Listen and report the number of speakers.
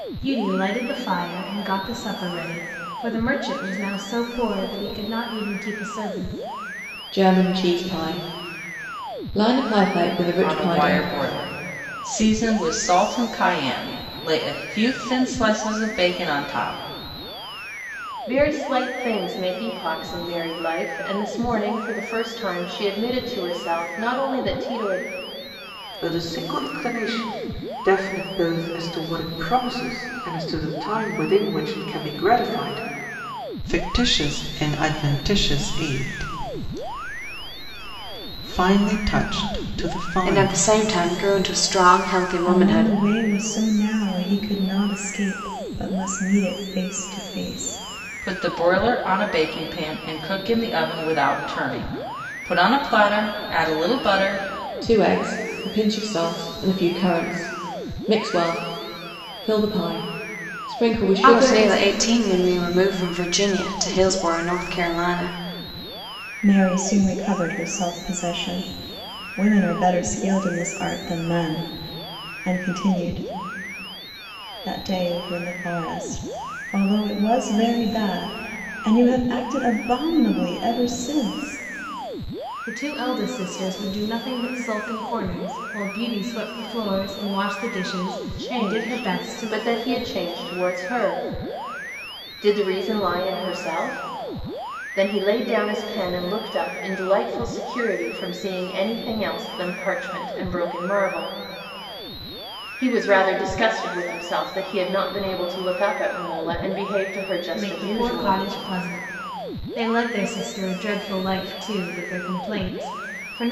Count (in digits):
8